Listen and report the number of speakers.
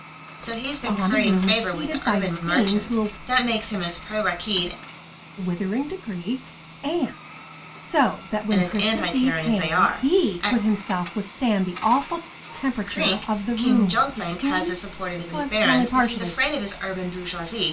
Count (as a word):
two